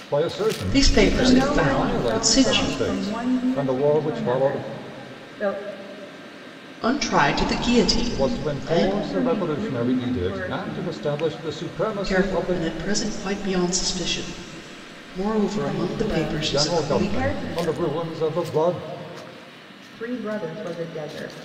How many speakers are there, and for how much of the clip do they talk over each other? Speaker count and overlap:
three, about 47%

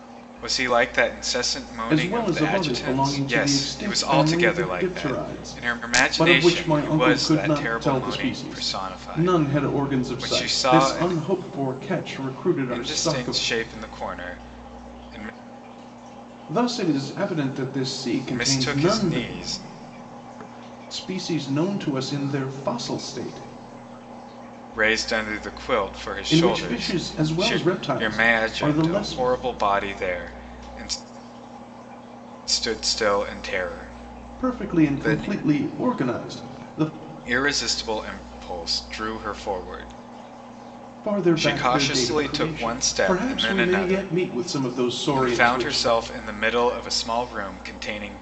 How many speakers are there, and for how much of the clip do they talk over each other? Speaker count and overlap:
two, about 37%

